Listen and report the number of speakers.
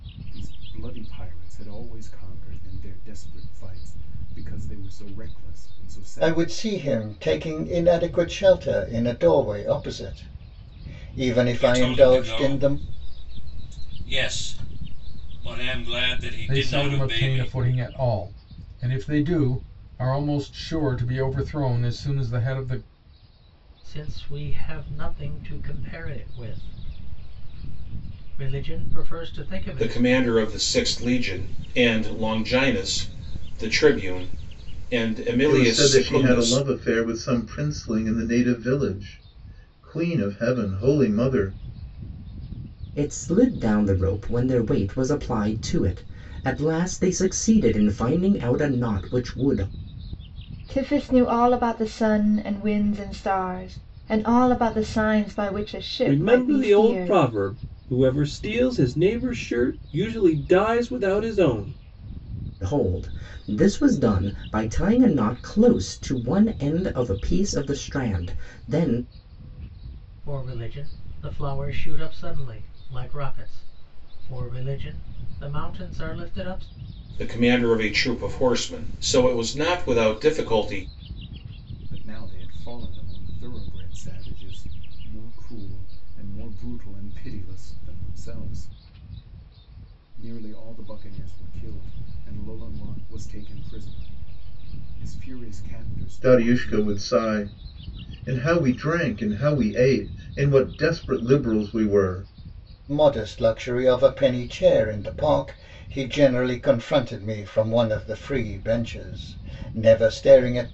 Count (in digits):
10